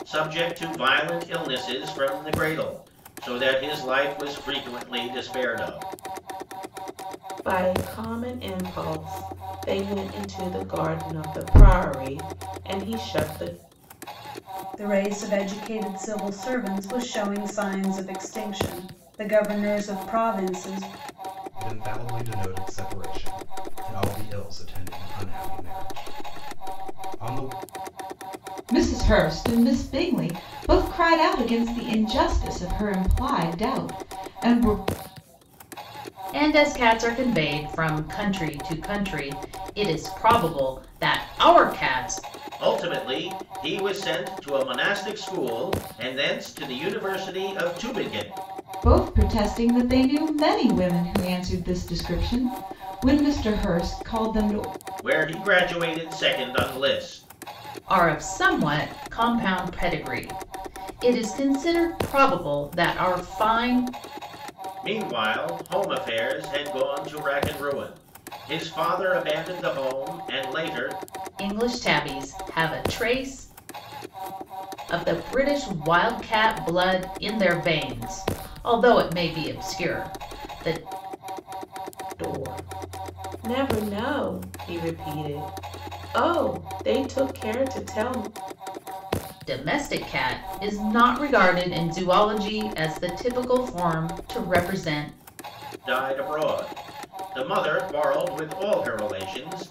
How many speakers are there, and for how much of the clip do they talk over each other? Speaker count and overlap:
6, no overlap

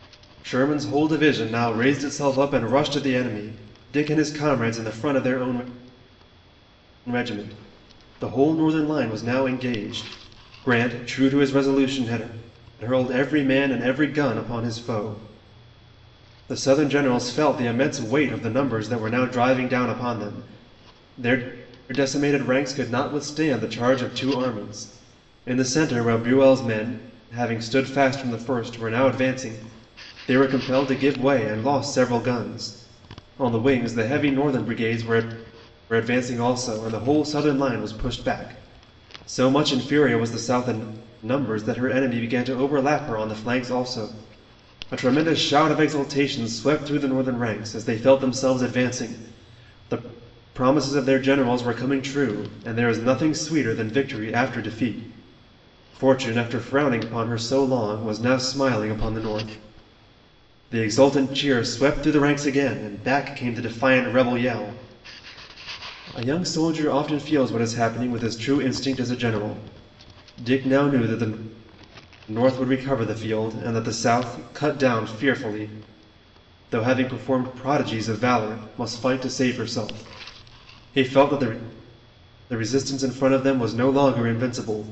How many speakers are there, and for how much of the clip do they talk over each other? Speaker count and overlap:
1, no overlap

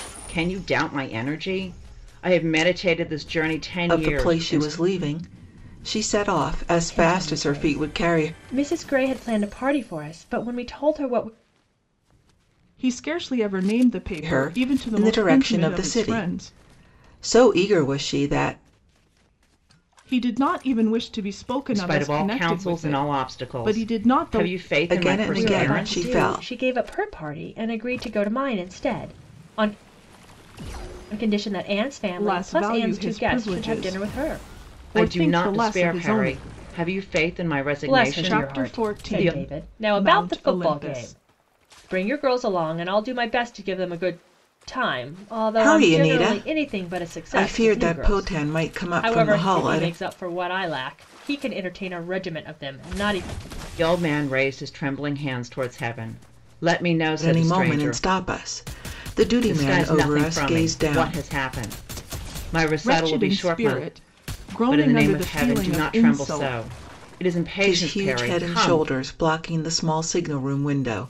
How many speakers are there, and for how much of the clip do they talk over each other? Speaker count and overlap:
4, about 38%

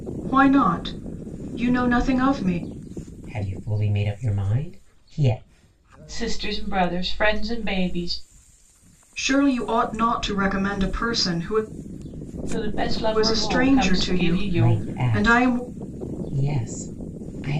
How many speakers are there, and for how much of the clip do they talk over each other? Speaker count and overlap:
3, about 14%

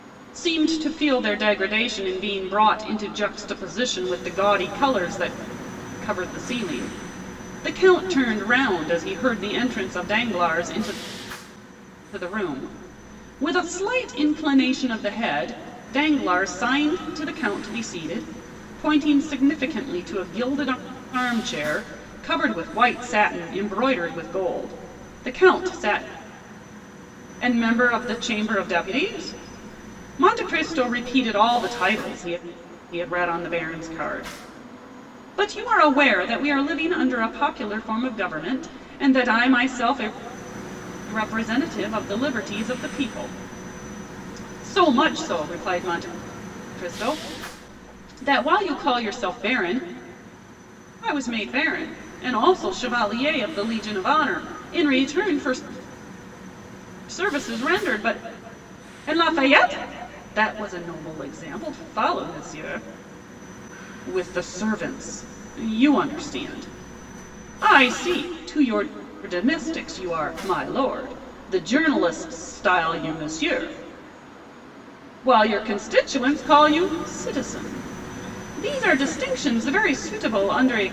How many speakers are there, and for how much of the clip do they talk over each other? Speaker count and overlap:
1, no overlap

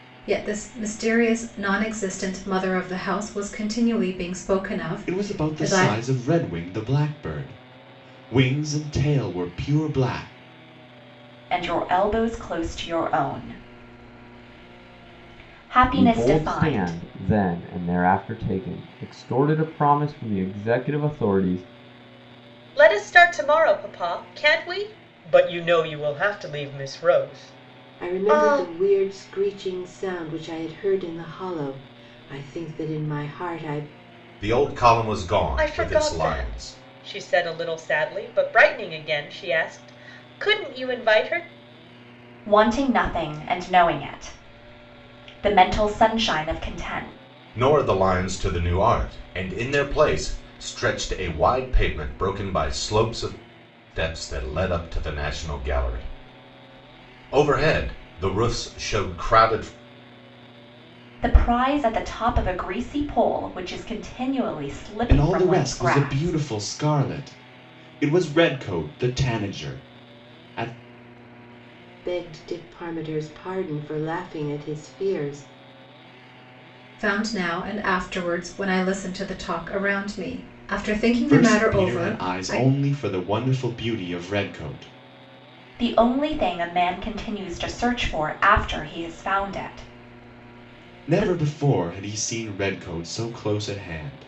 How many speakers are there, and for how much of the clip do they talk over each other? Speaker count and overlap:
7, about 8%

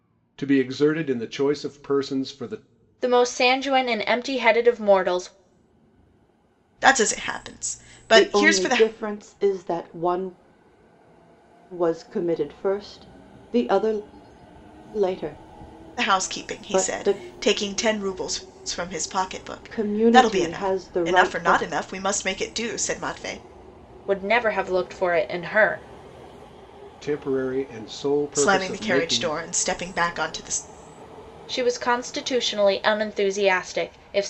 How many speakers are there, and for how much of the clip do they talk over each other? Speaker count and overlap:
4, about 14%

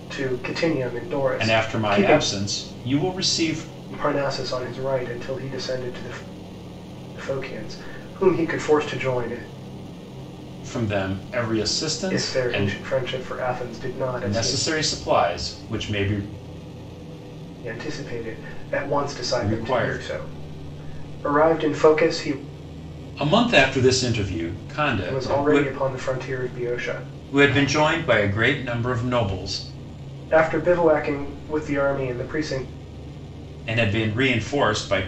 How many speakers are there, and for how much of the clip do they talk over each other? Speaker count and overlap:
2, about 9%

